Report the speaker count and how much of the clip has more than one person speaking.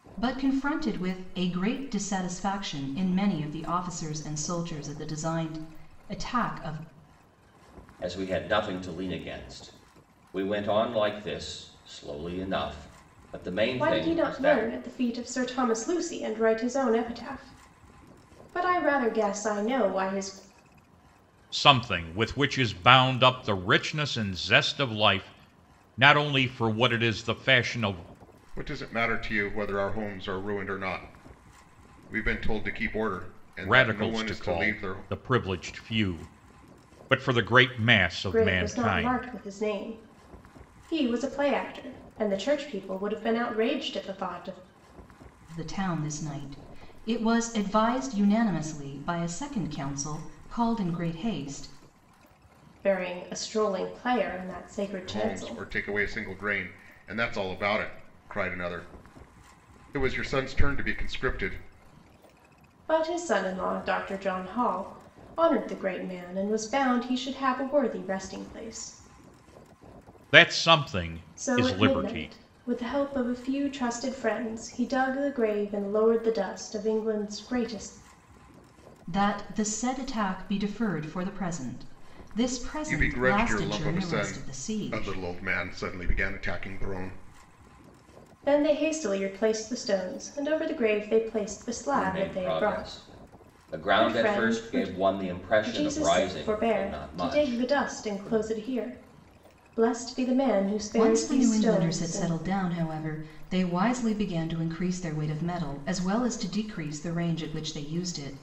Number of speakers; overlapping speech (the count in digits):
5, about 13%